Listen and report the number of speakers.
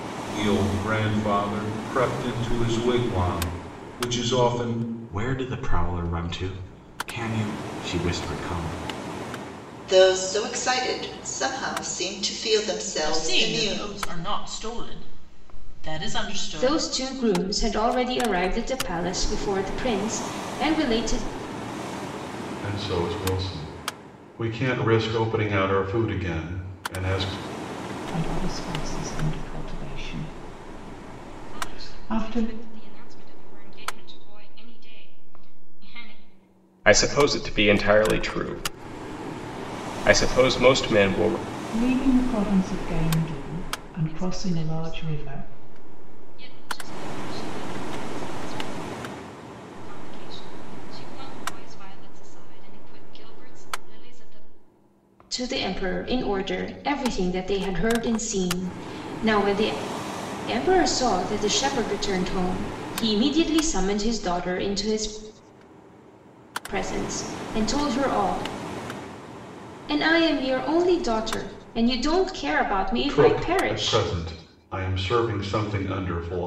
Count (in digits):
9